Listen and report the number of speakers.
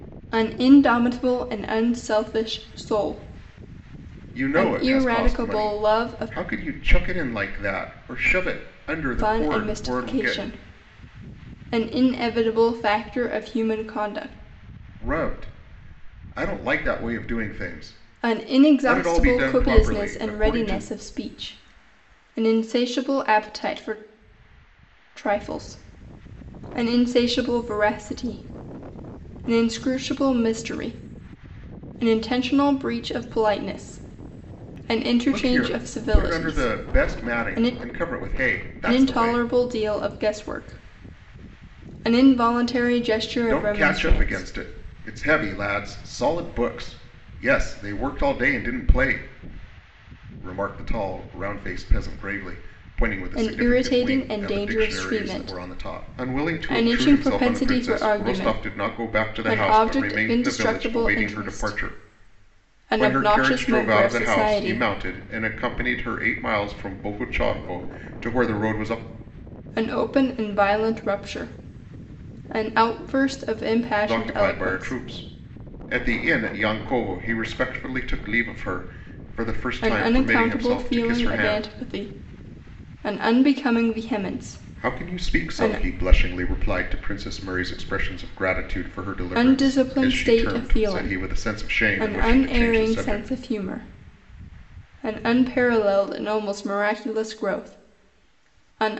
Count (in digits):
2